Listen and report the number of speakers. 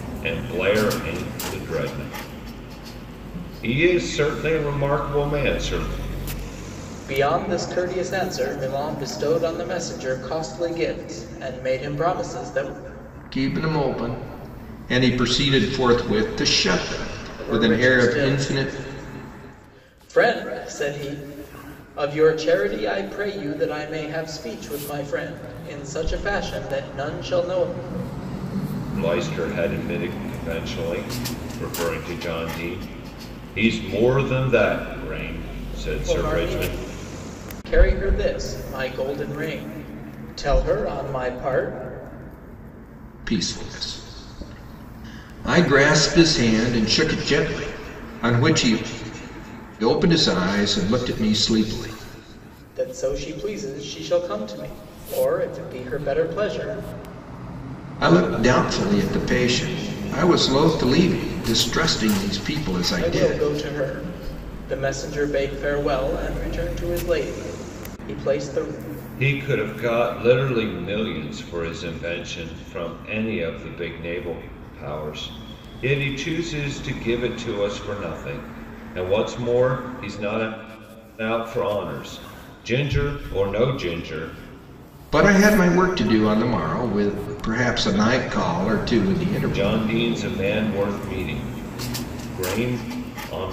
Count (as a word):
three